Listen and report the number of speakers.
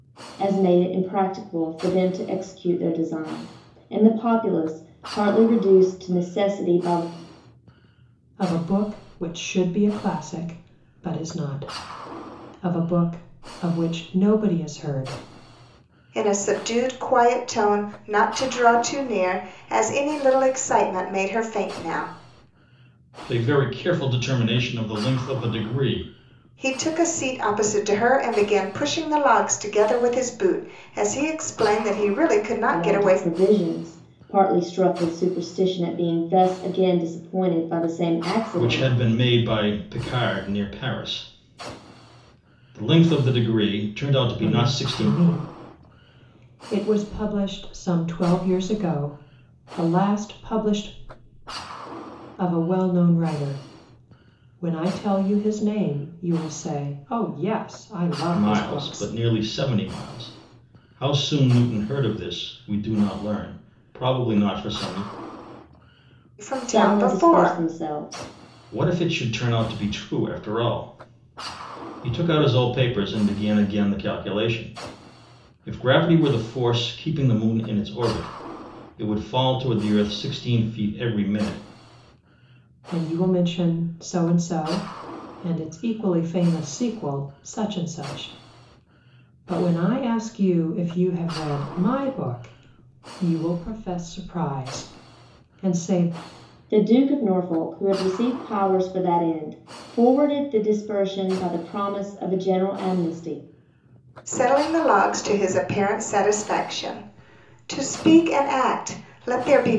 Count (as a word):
four